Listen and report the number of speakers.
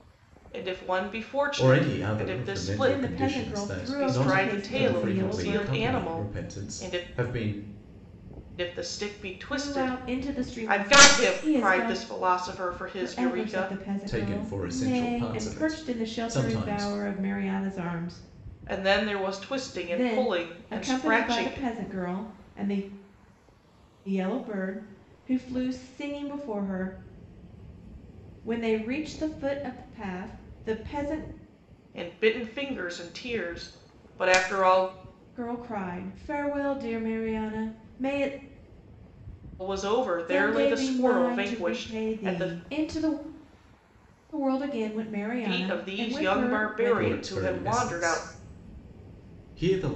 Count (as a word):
three